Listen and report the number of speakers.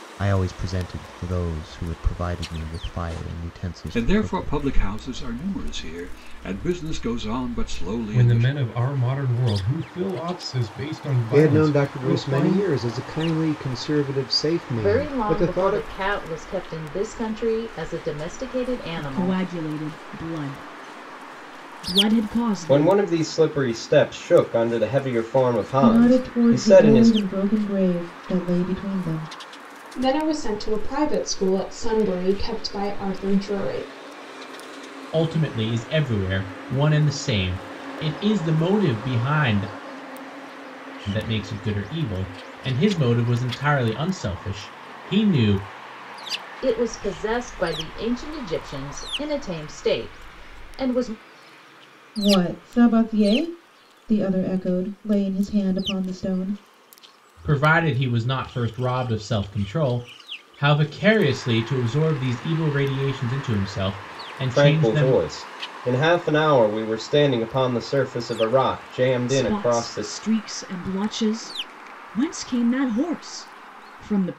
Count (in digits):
10